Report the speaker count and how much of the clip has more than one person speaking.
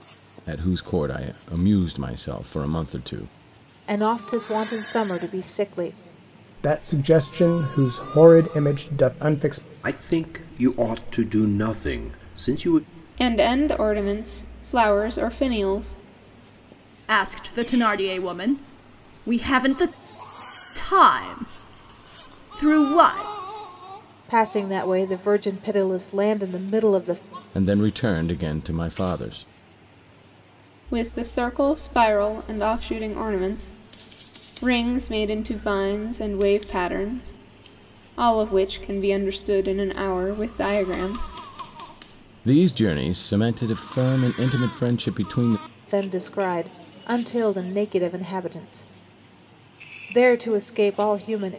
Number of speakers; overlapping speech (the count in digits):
6, no overlap